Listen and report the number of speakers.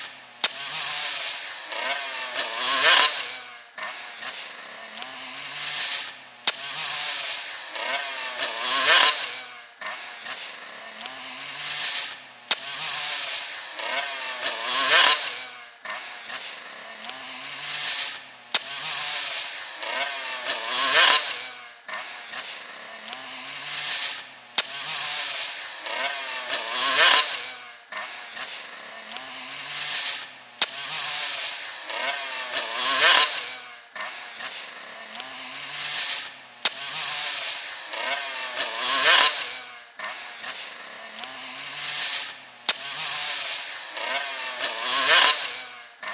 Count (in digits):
0